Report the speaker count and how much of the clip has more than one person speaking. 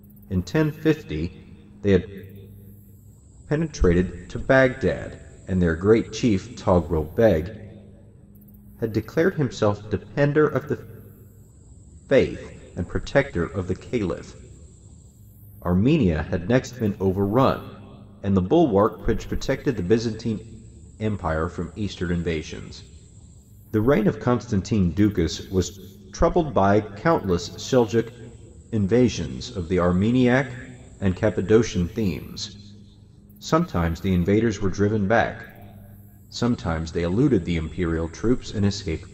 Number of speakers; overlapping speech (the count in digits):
1, no overlap